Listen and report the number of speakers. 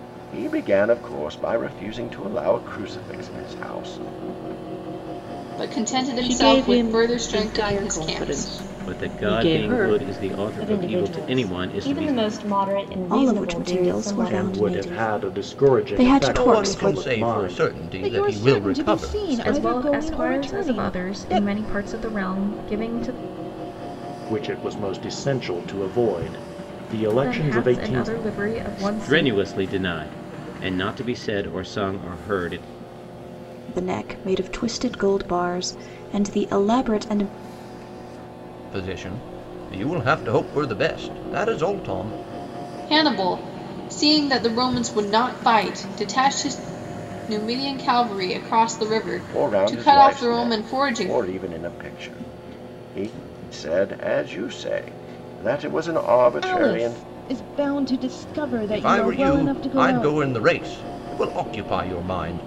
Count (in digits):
10